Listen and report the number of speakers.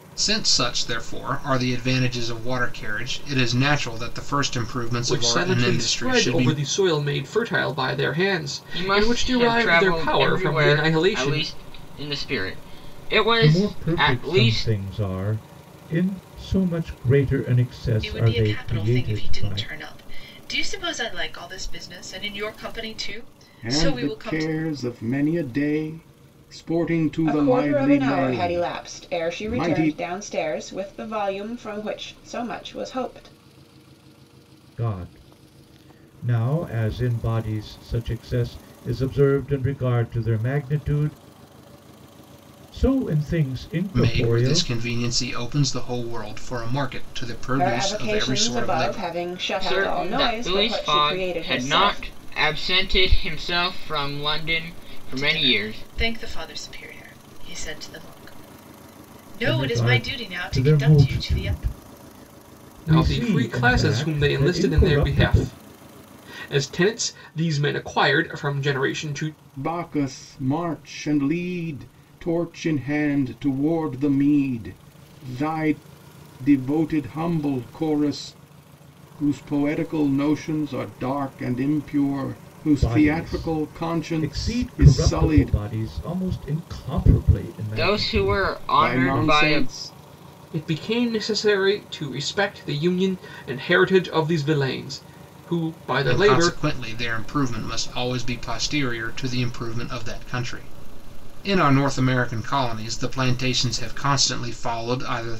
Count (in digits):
7